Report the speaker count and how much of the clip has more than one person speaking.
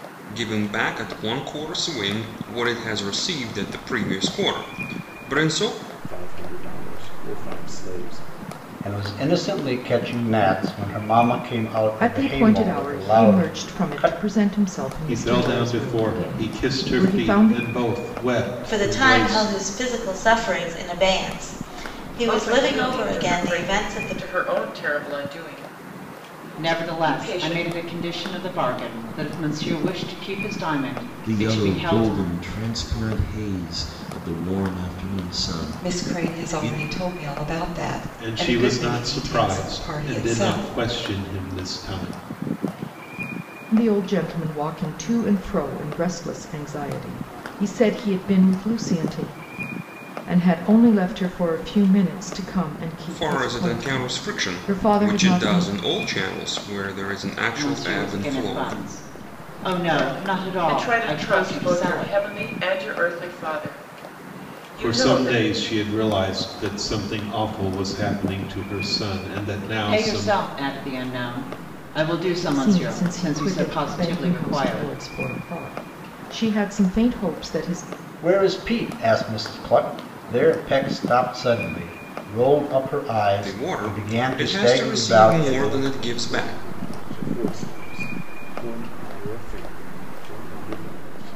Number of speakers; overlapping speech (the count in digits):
10, about 30%